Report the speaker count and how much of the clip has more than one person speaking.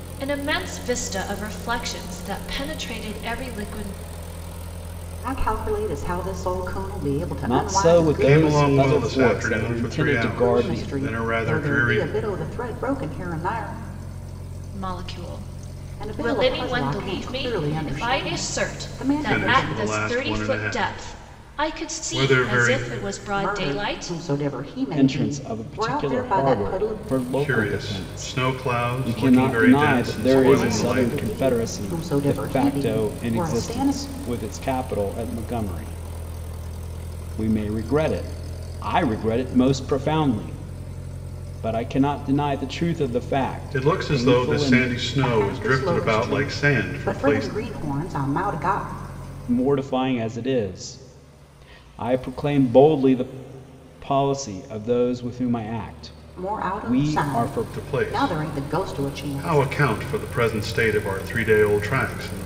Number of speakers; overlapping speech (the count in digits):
4, about 44%